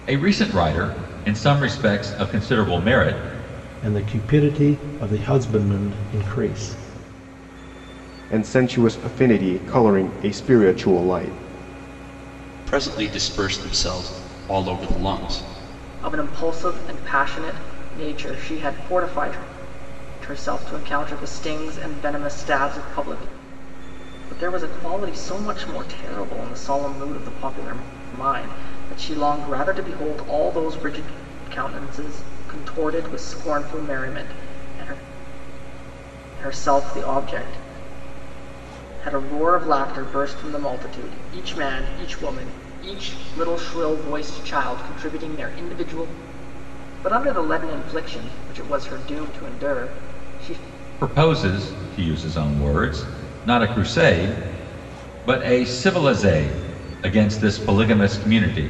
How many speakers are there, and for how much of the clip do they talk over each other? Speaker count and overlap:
5, no overlap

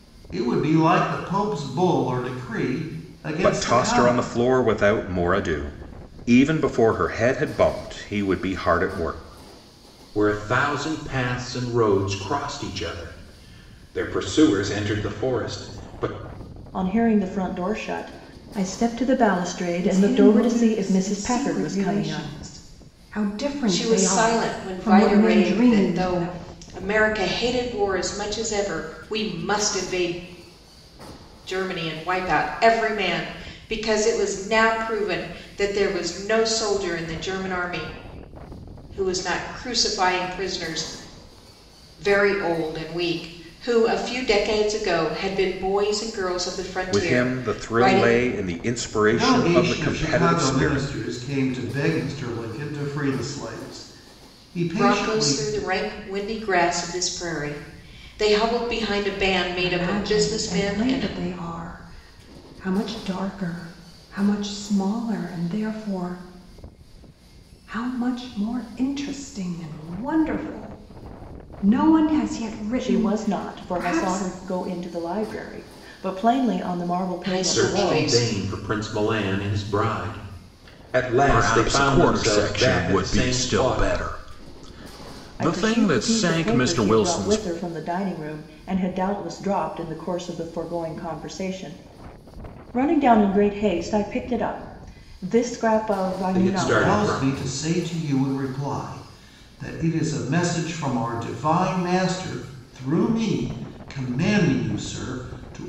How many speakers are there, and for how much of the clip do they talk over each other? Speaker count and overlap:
6, about 21%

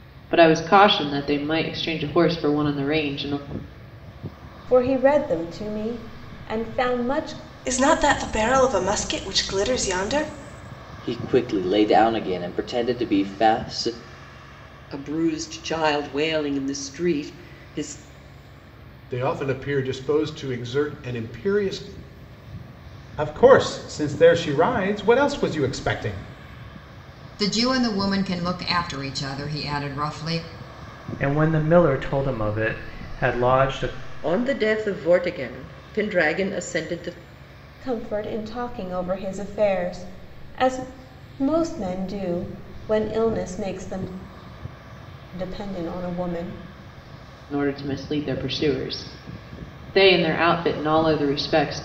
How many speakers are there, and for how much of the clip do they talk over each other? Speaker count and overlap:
10, no overlap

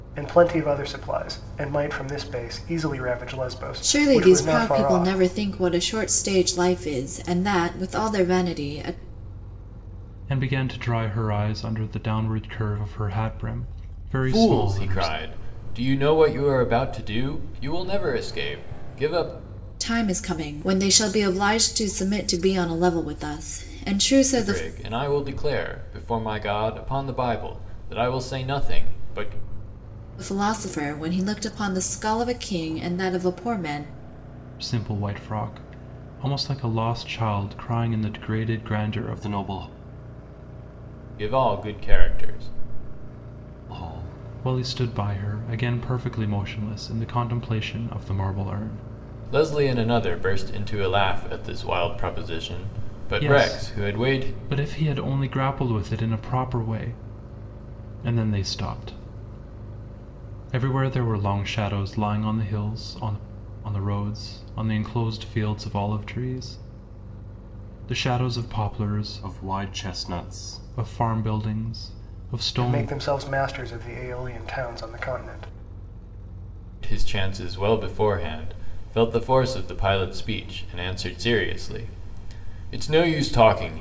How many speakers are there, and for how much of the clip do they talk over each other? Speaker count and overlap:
4, about 5%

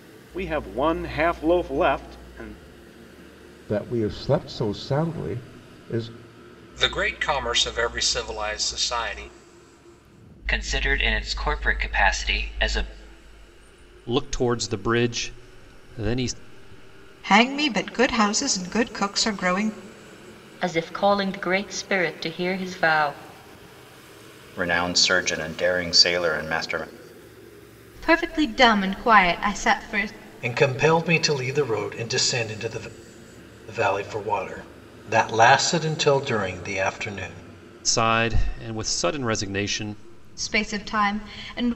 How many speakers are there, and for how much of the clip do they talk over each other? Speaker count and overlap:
10, no overlap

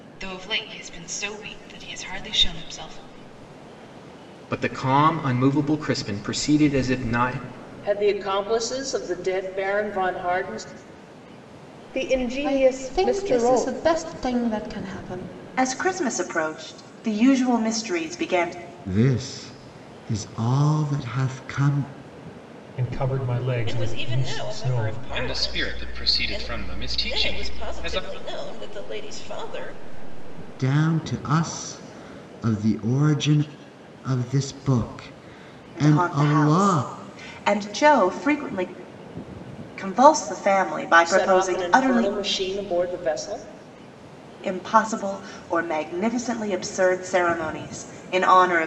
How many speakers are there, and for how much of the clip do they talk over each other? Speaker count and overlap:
10, about 15%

